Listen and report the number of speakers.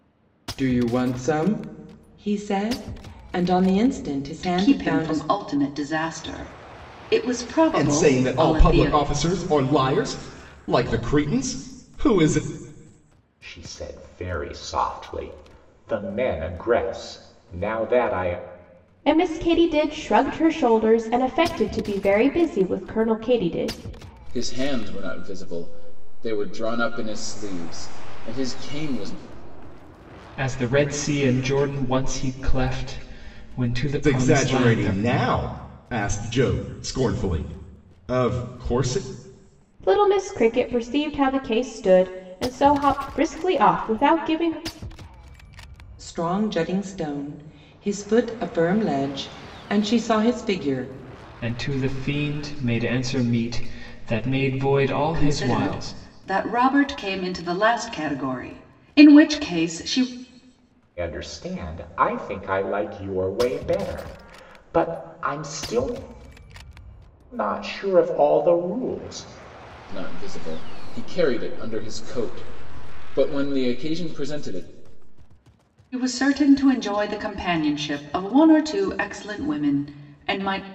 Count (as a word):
seven